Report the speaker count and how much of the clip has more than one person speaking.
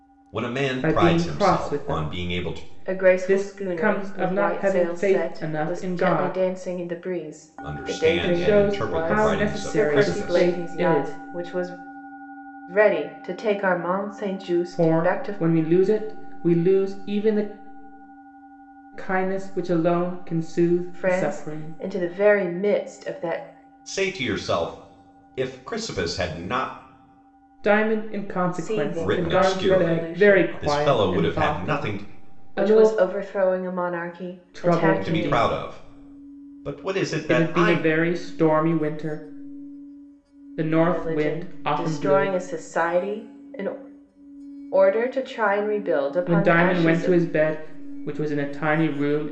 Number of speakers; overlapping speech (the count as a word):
three, about 38%